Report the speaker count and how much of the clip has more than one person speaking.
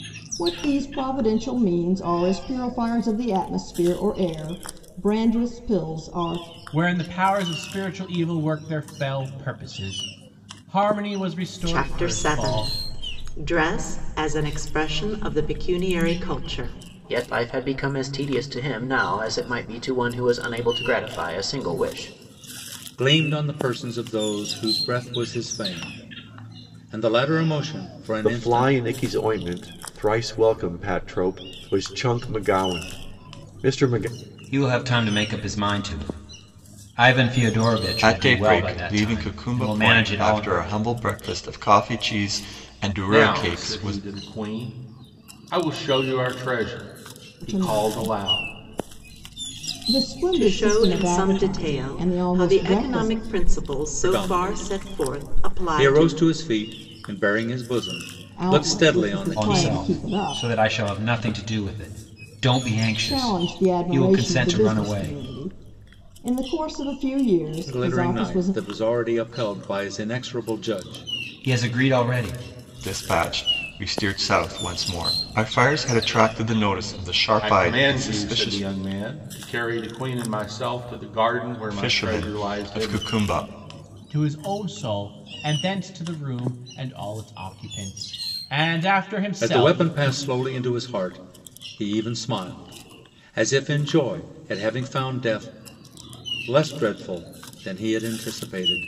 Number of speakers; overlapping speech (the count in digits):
9, about 20%